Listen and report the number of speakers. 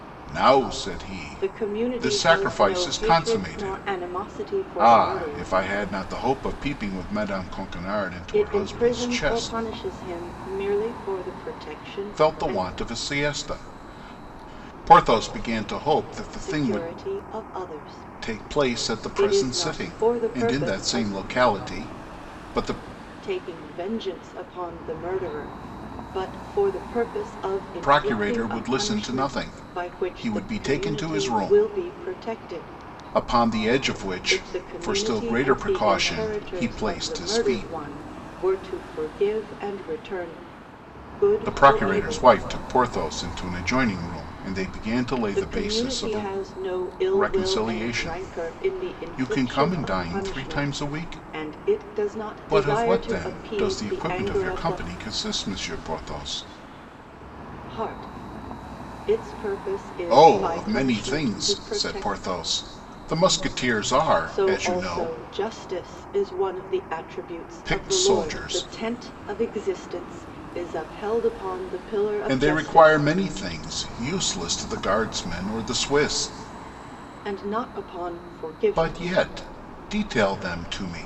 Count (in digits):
2